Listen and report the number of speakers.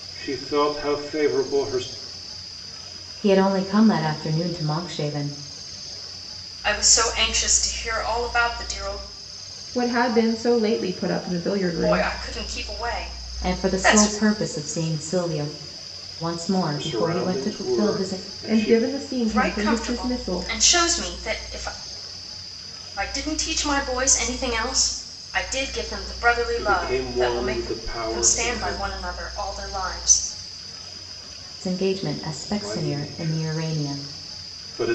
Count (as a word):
four